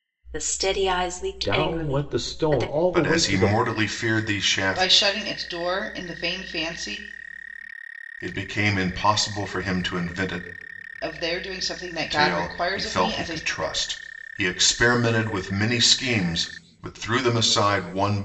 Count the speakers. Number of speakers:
four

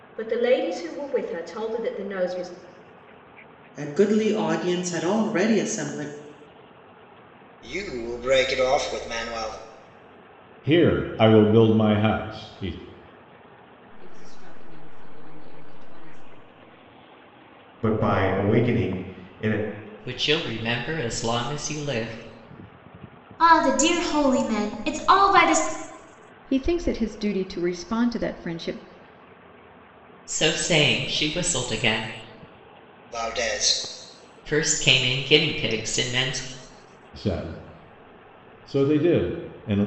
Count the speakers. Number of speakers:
nine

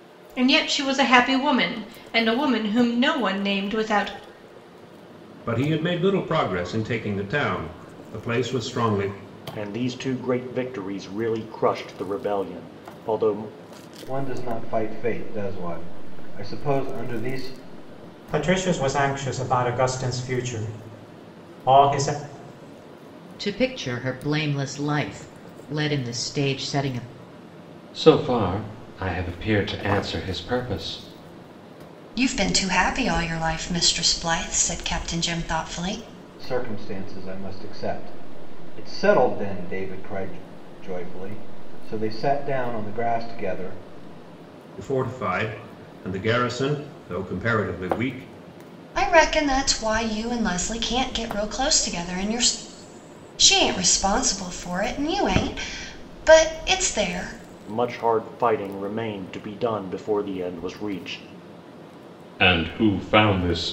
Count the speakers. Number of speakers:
eight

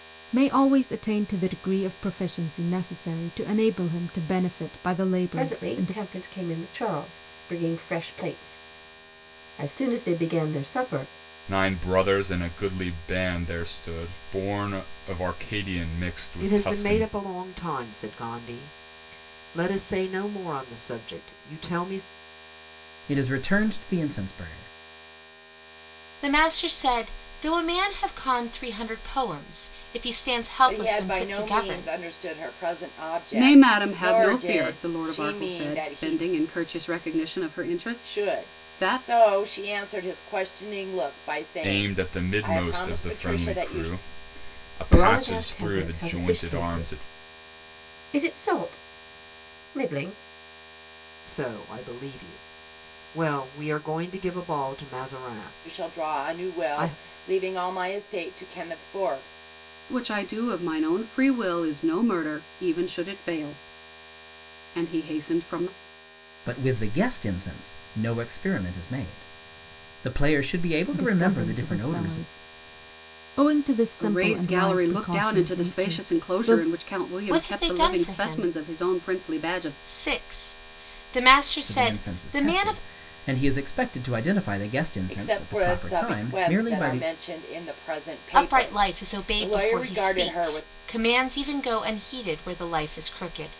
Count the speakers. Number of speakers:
eight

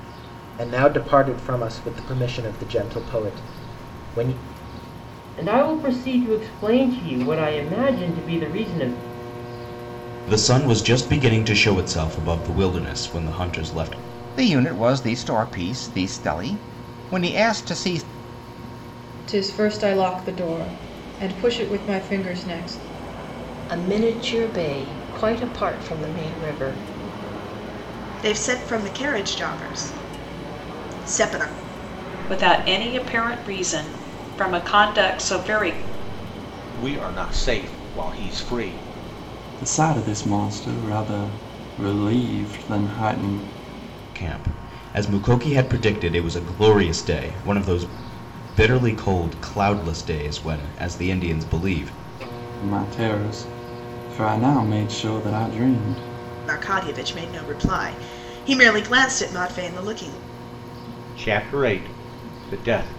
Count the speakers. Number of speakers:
ten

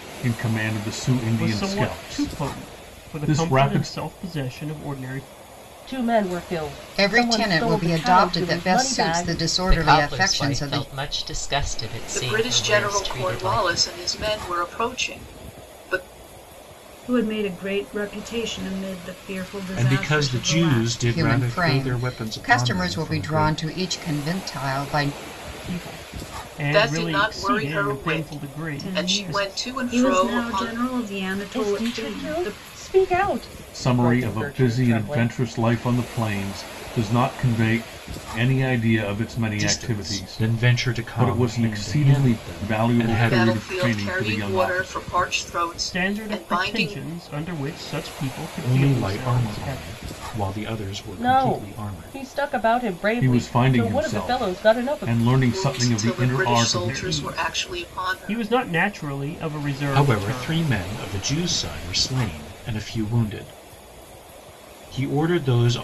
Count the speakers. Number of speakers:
eight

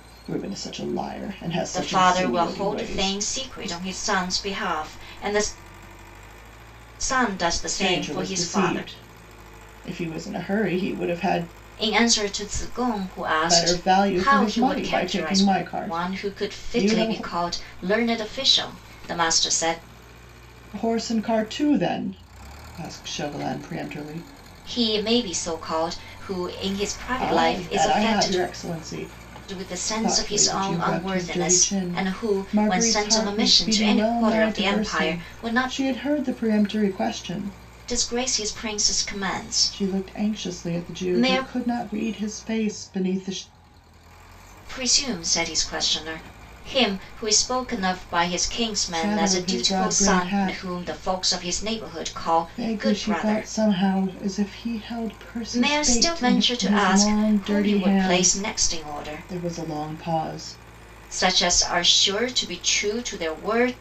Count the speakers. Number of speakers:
two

